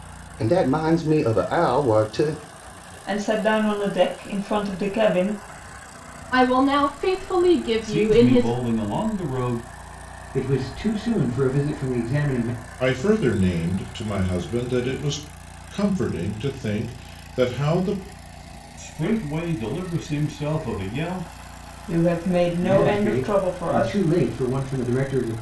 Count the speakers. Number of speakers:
6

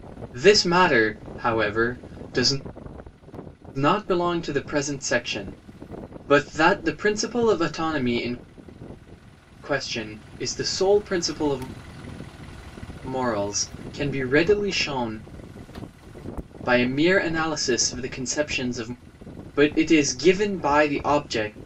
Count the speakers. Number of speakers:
1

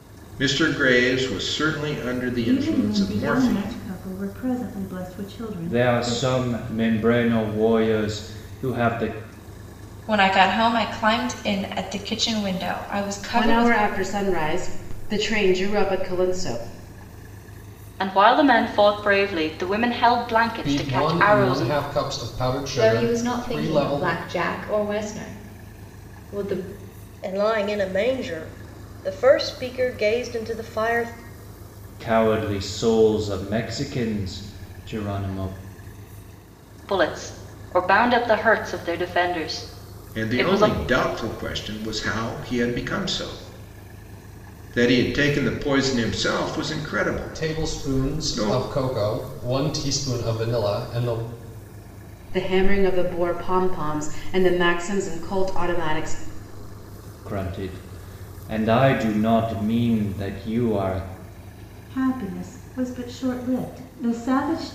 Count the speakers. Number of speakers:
9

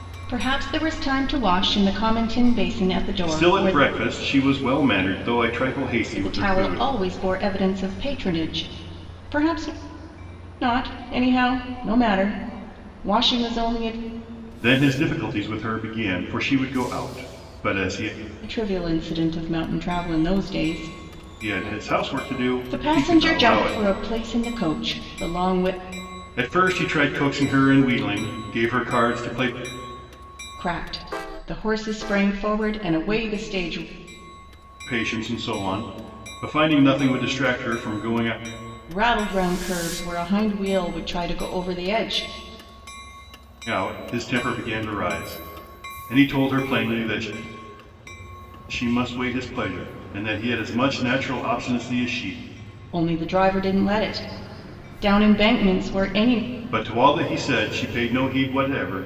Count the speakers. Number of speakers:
2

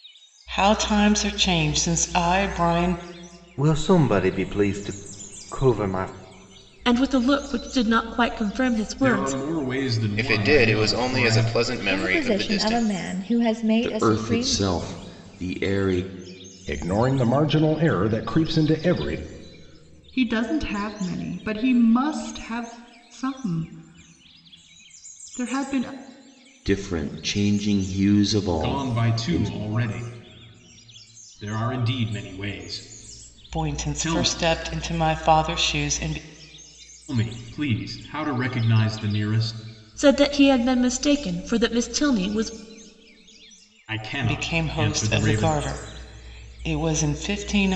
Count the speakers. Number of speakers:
9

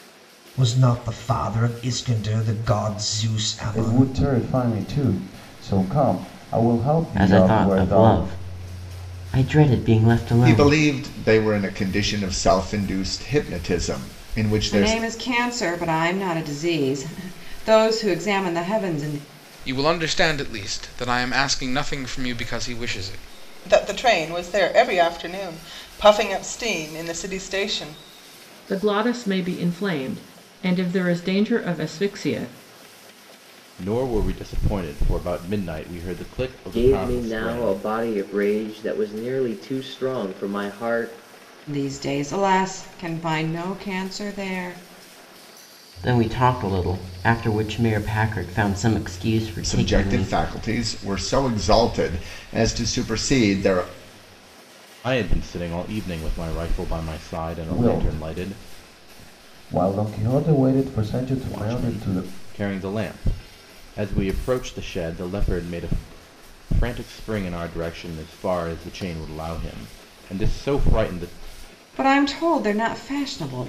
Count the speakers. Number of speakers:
10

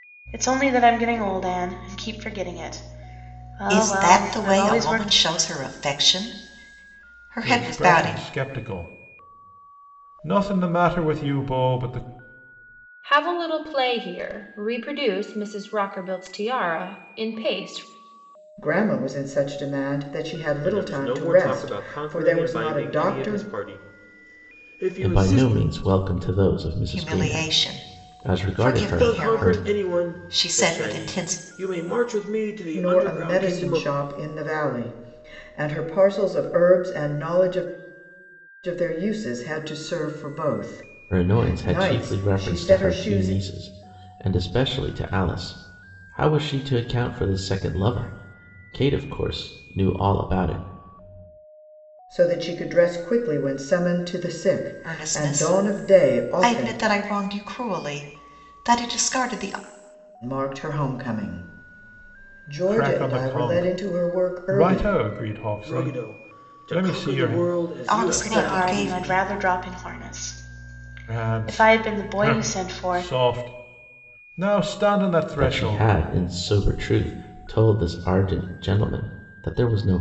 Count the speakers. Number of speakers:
7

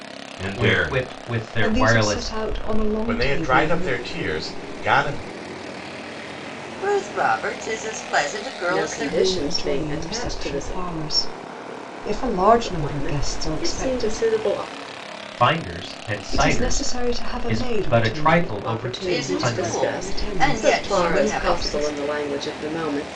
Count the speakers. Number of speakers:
6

